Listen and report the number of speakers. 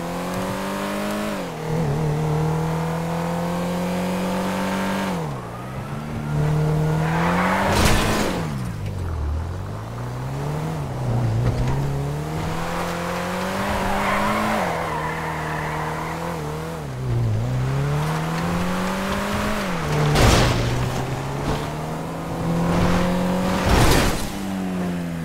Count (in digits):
0